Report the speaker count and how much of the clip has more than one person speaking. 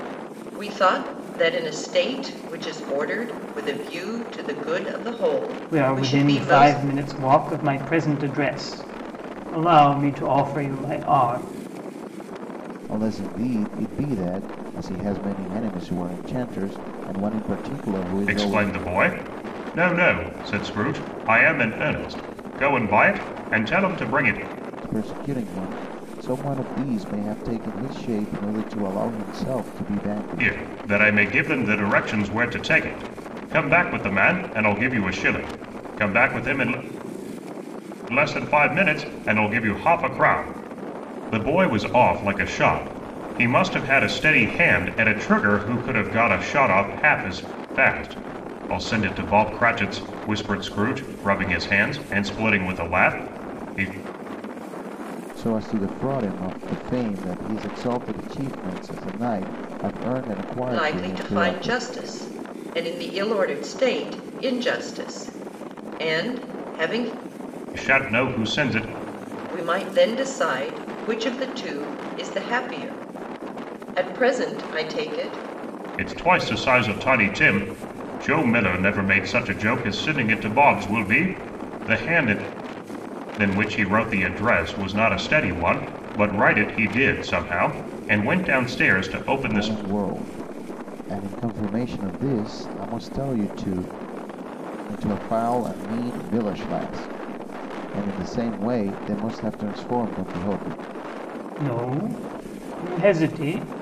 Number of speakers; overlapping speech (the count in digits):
4, about 3%